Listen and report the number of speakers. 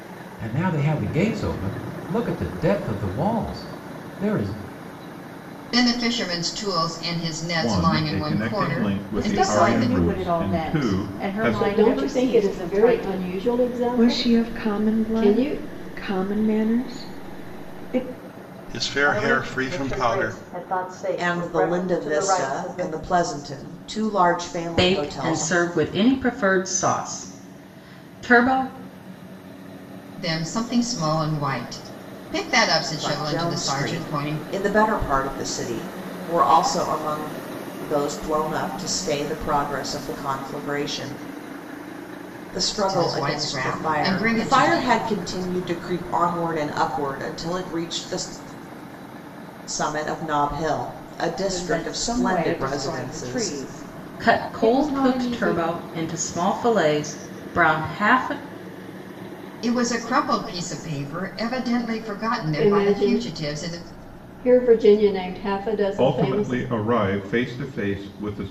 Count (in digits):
10